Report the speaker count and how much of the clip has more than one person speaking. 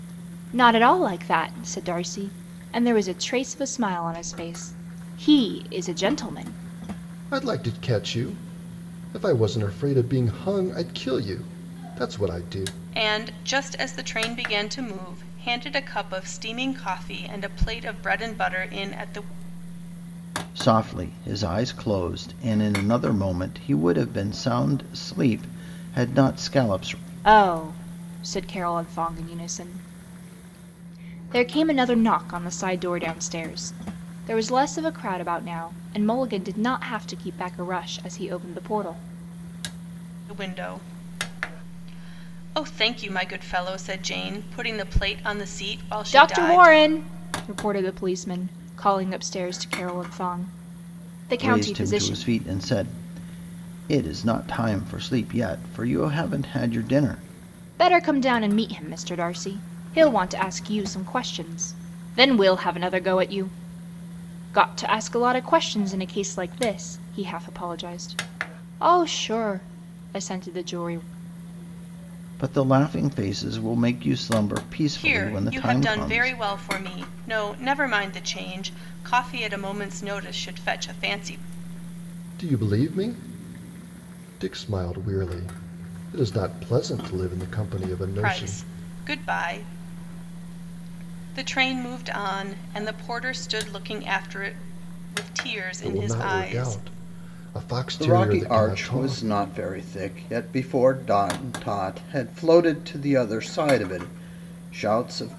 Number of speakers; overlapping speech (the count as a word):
four, about 6%